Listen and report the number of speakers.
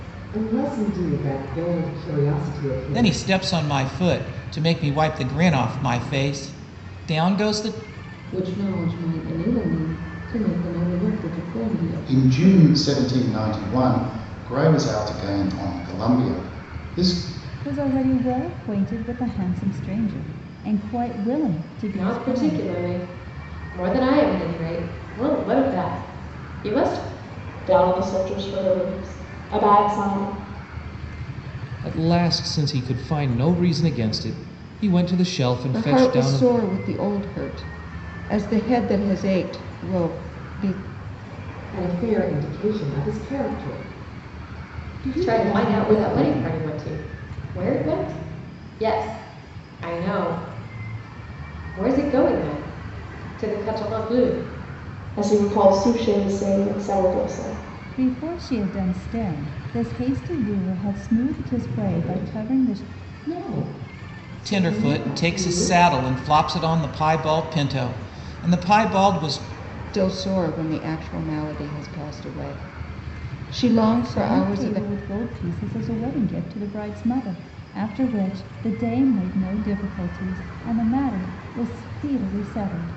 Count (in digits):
9